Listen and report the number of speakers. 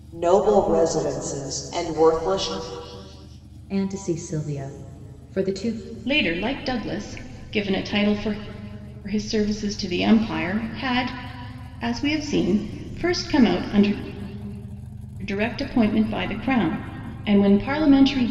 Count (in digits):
3